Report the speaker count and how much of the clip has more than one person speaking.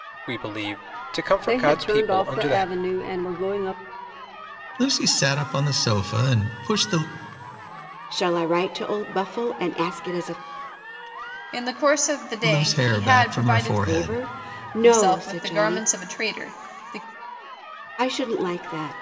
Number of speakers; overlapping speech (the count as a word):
five, about 22%